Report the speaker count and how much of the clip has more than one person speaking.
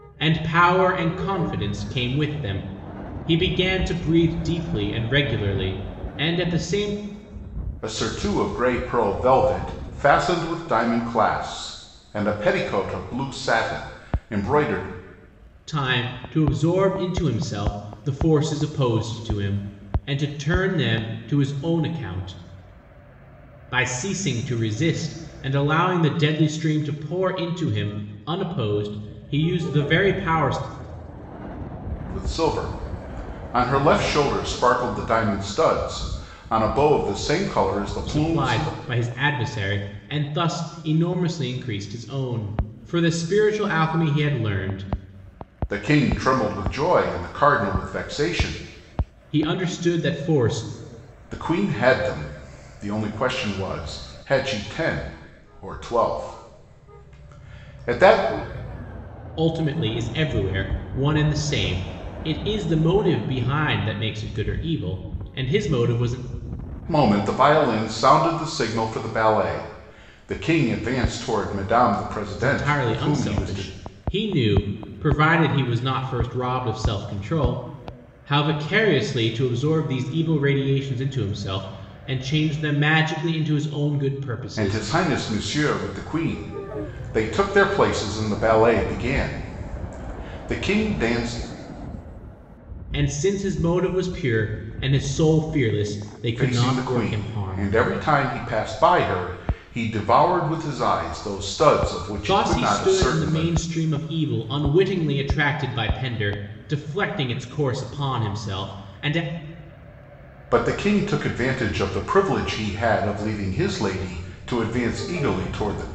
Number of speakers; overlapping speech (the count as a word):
two, about 4%